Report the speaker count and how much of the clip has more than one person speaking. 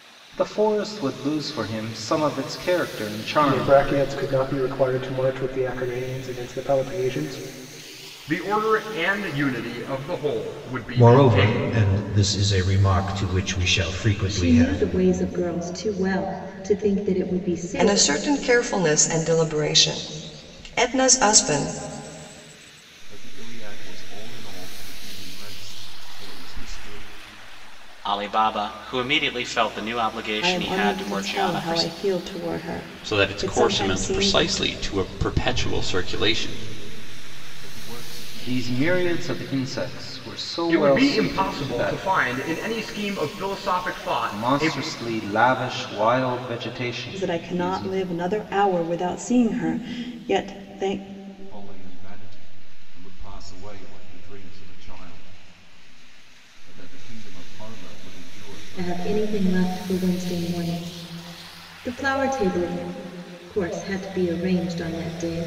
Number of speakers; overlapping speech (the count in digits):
10, about 17%